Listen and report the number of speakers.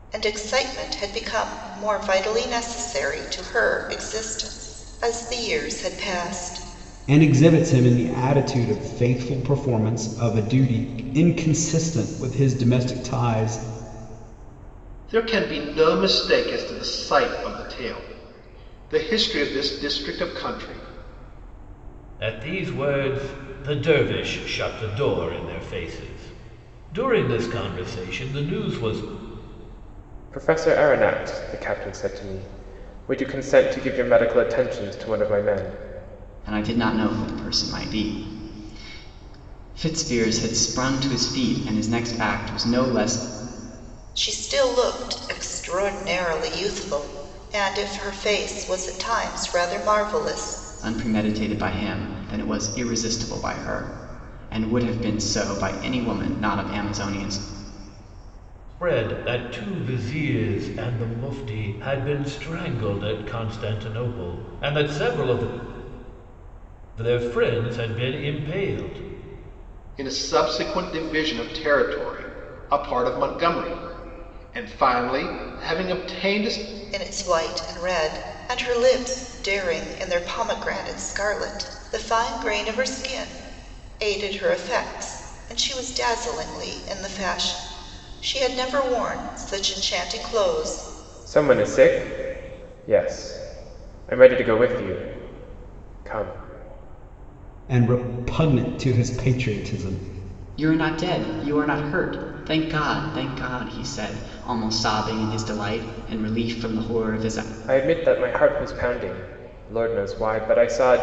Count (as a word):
six